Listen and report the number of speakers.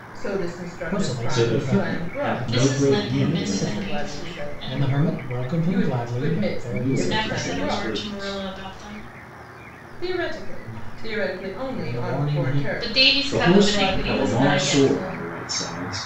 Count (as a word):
four